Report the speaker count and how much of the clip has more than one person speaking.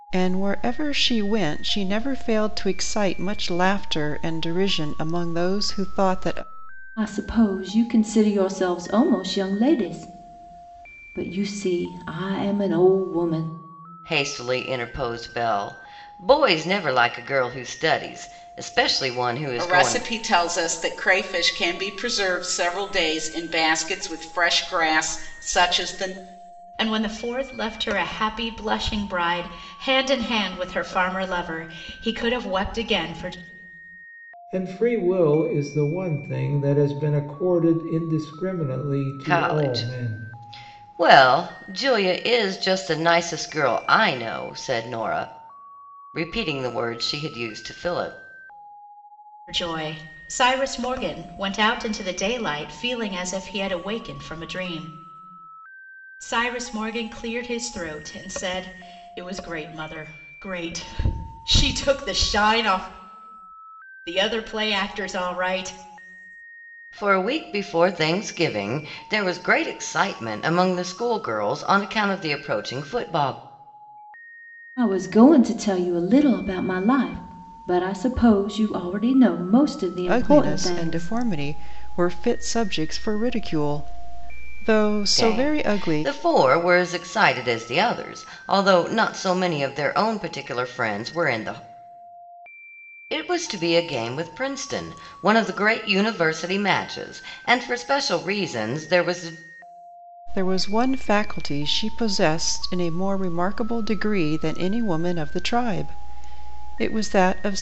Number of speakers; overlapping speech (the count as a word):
six, about 3%